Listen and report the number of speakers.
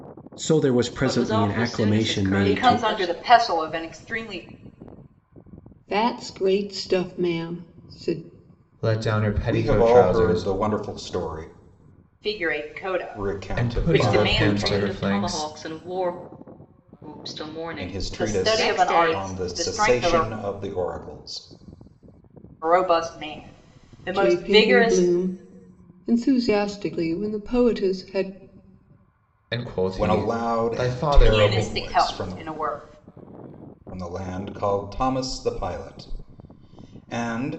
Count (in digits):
6